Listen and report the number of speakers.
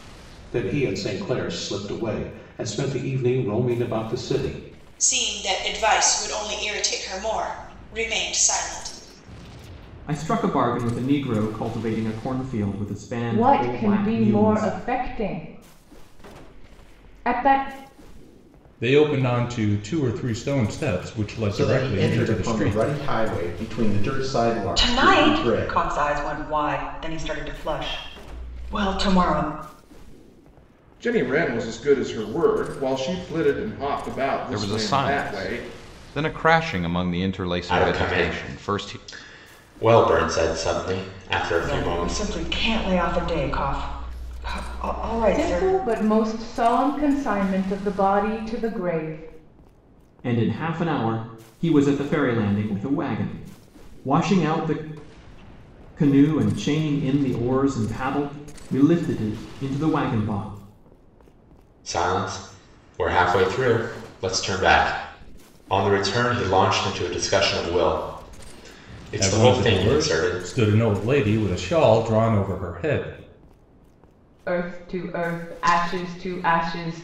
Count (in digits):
10